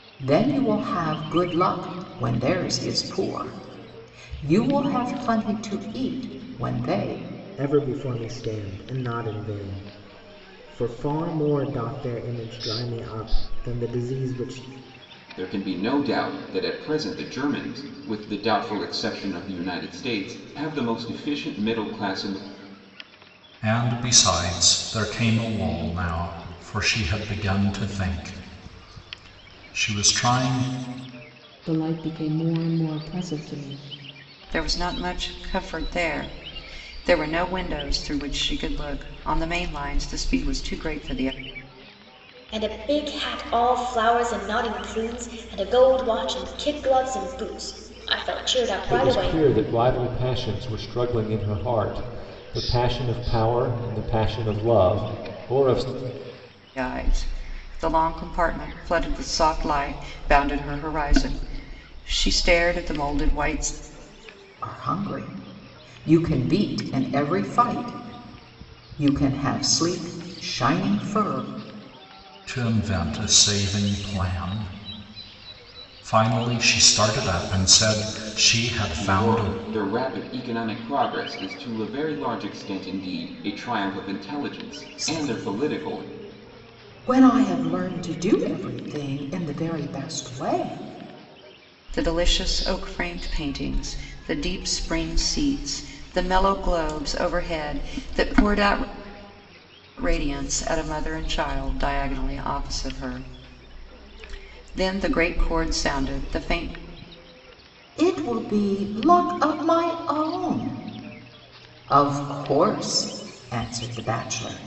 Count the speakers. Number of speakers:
8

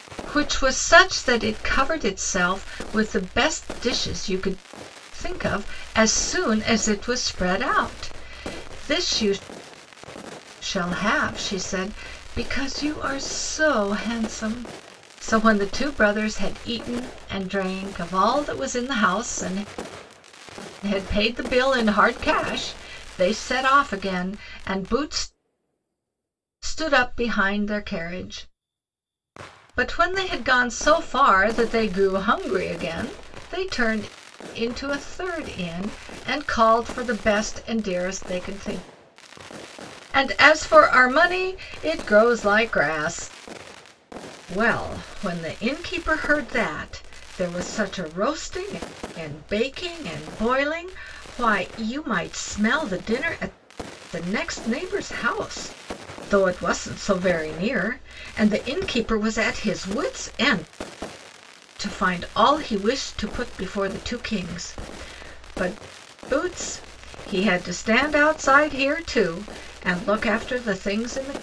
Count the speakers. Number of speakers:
1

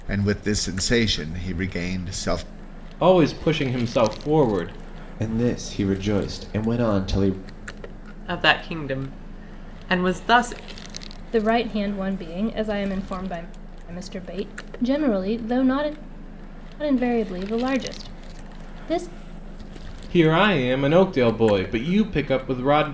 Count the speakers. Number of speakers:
5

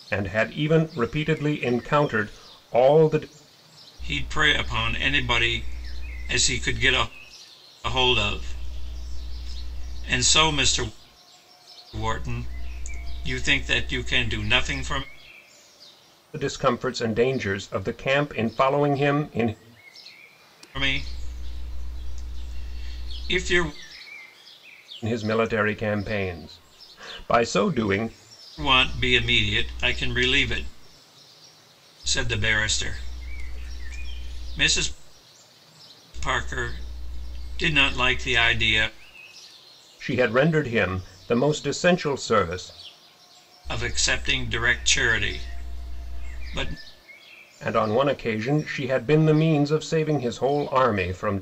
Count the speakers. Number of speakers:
2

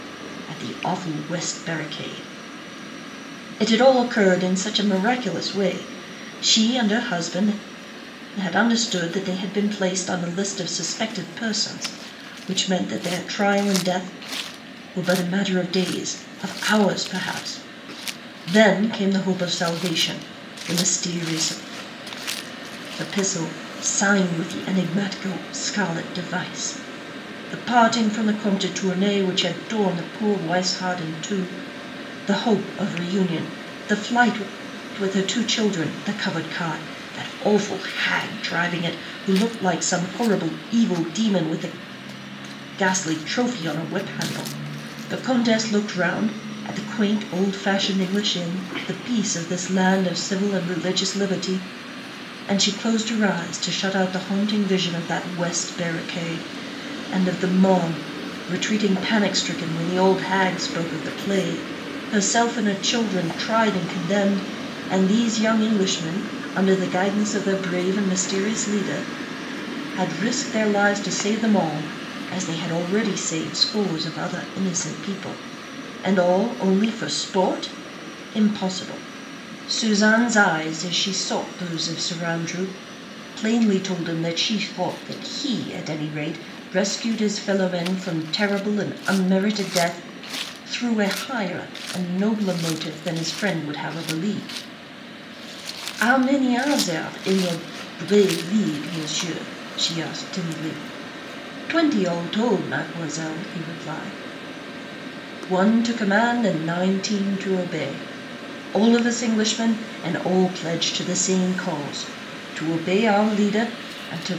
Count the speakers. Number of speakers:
1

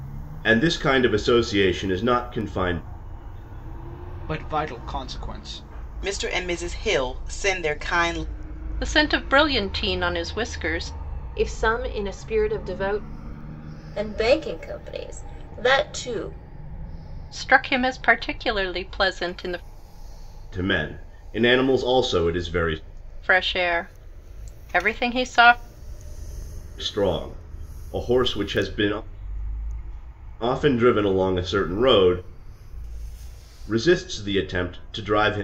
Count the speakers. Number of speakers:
6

